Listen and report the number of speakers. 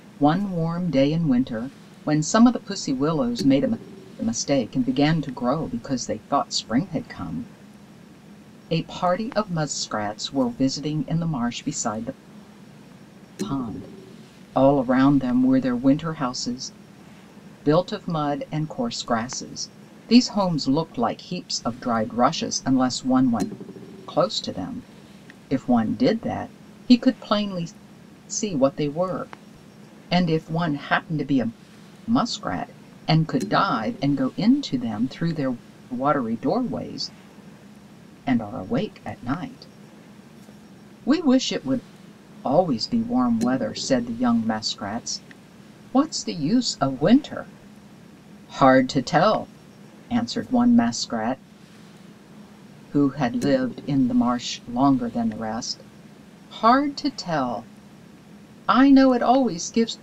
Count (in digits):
1